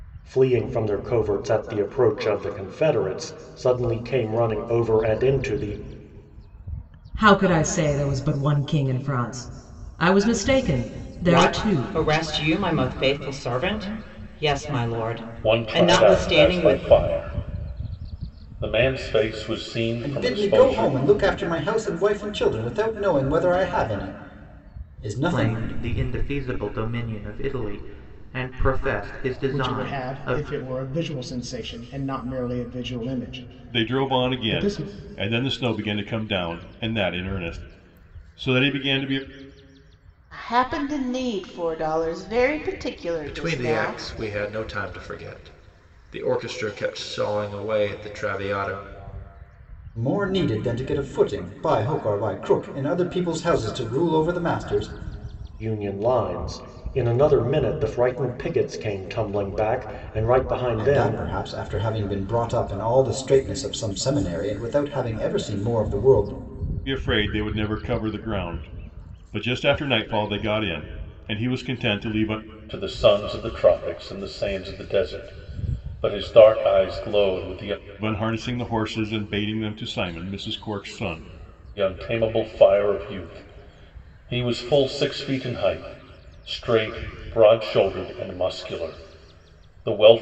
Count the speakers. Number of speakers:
ten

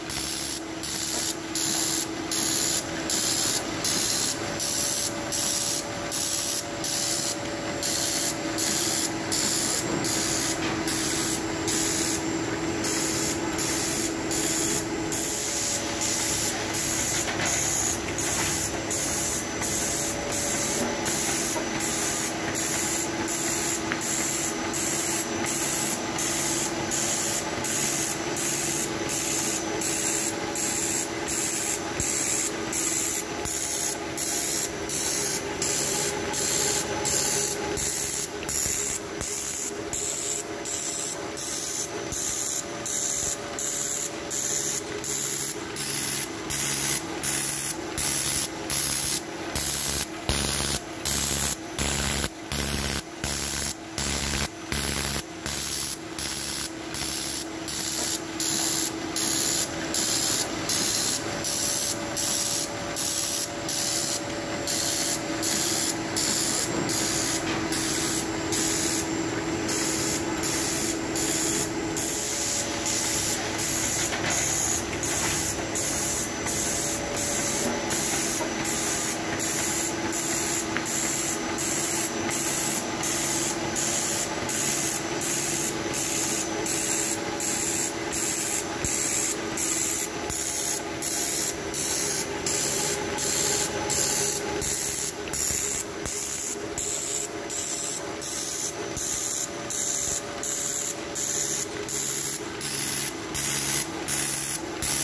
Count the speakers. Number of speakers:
zero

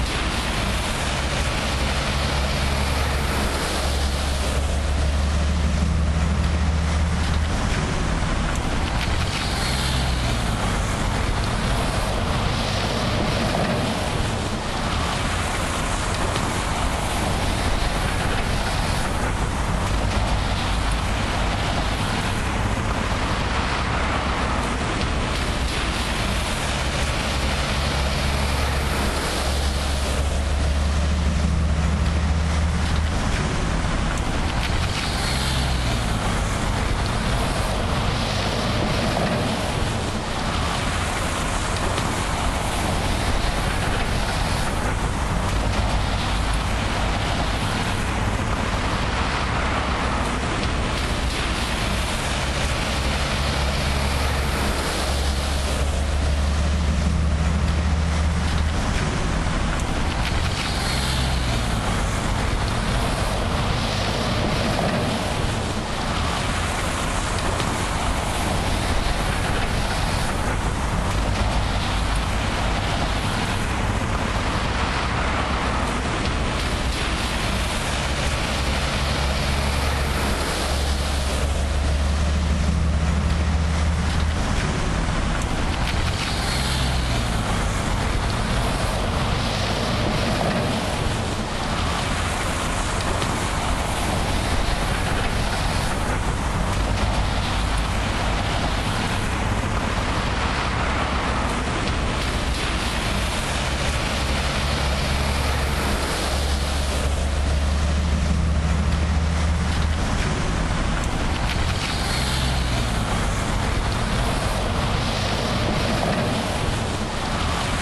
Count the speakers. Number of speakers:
zero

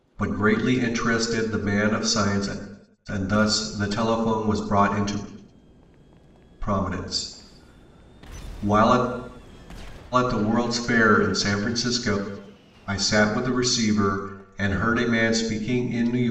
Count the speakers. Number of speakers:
one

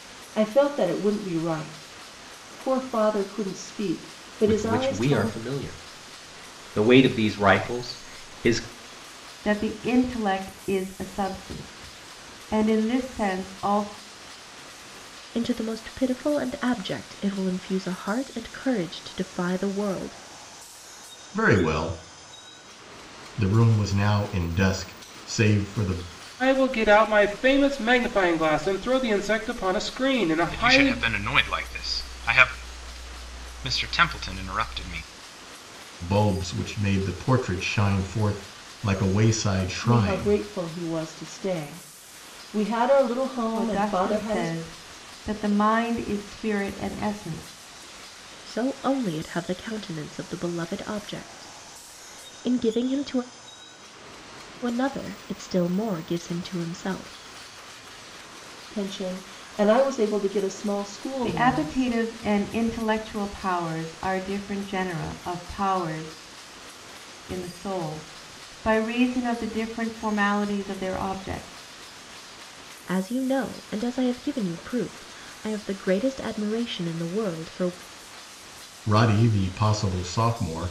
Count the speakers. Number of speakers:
seven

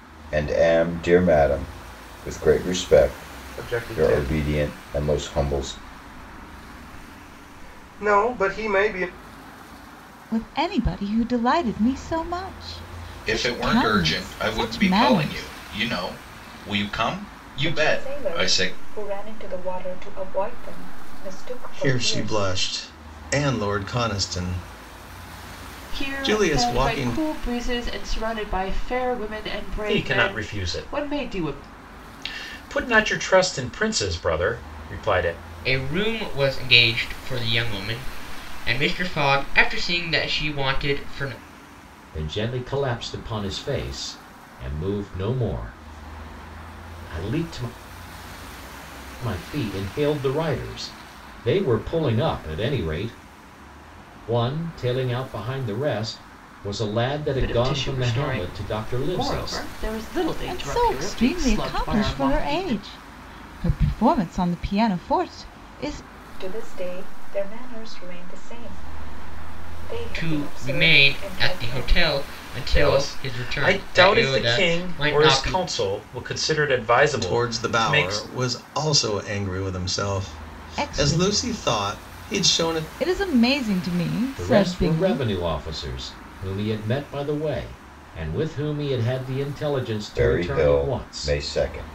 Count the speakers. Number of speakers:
ten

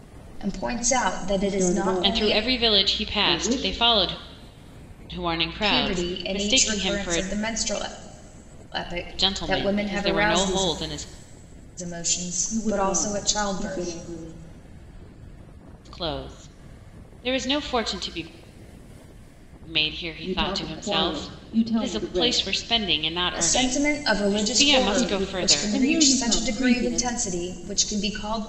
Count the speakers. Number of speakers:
three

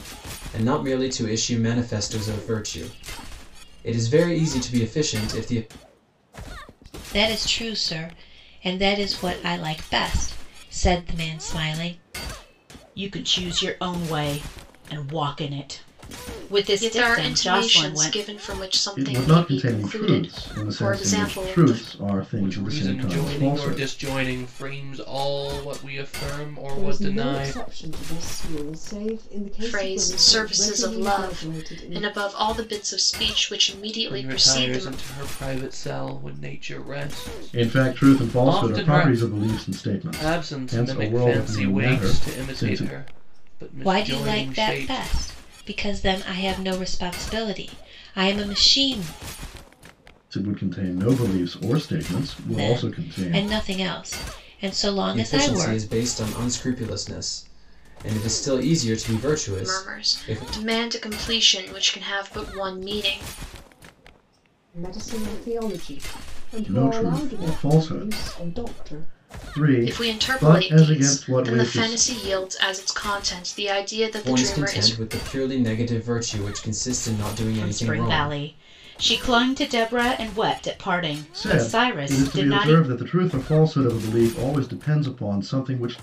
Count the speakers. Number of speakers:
seven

